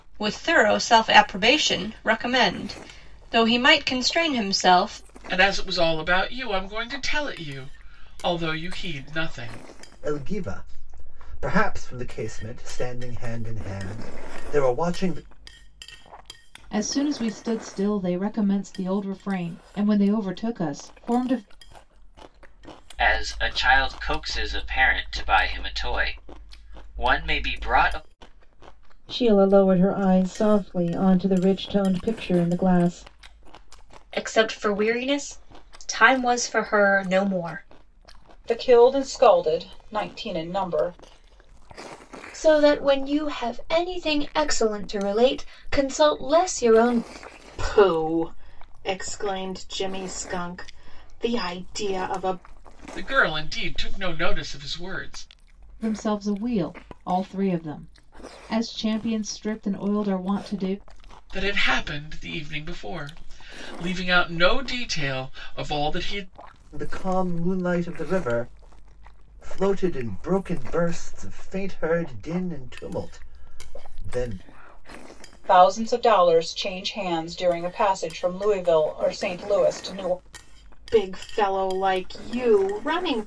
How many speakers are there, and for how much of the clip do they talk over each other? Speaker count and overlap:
10, no overlap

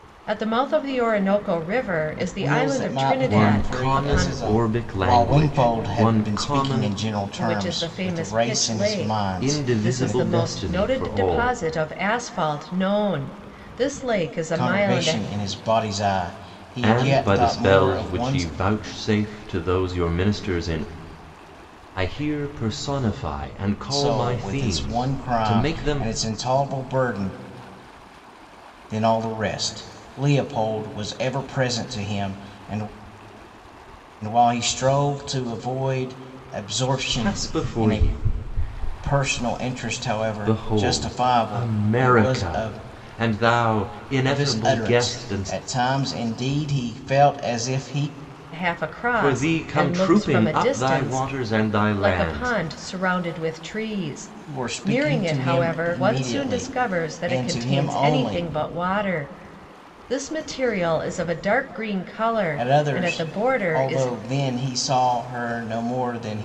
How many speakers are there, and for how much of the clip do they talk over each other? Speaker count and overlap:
3, about 42%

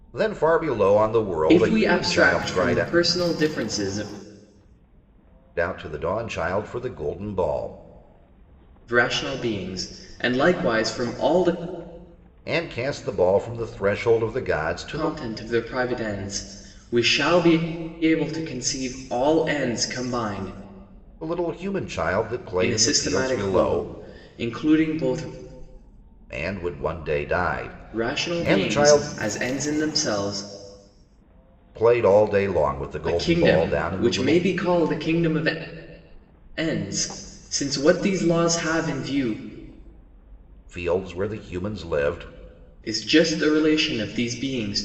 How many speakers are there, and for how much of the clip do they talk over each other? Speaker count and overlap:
2, about 13%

